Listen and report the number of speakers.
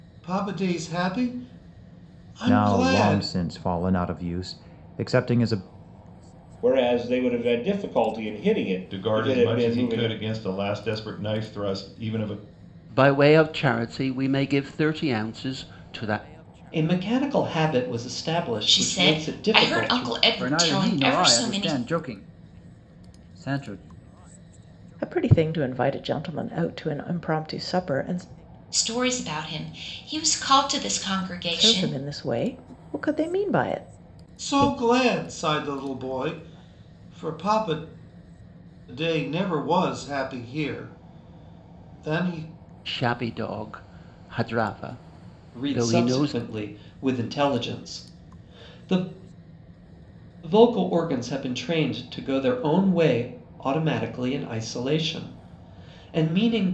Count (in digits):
9